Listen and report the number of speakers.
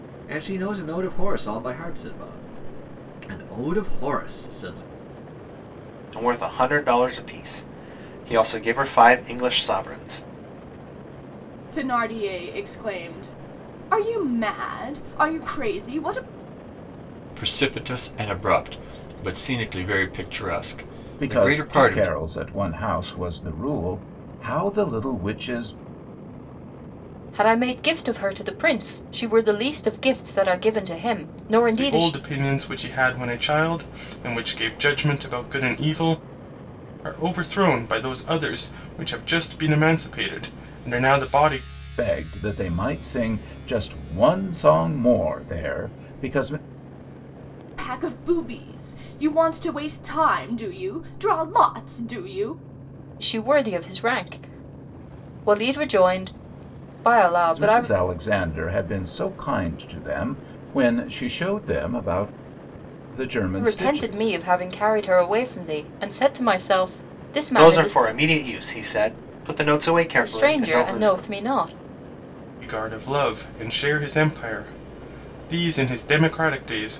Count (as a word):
seven